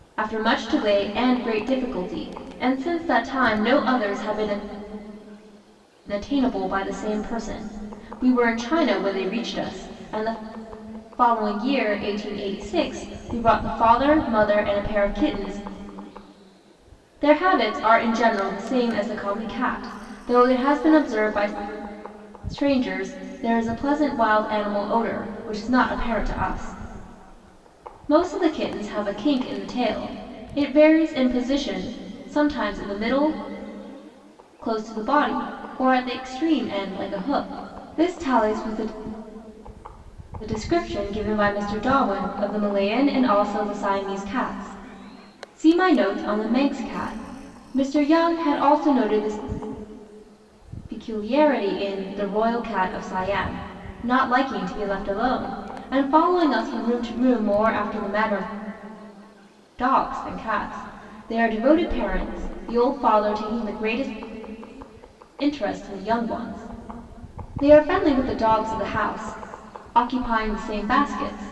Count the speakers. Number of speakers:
one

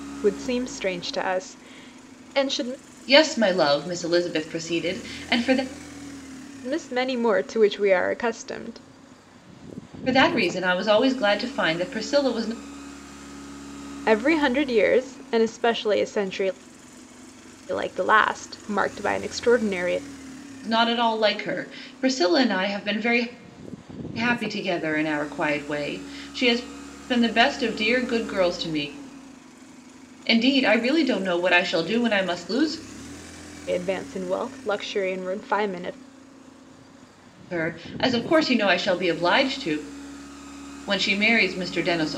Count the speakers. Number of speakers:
two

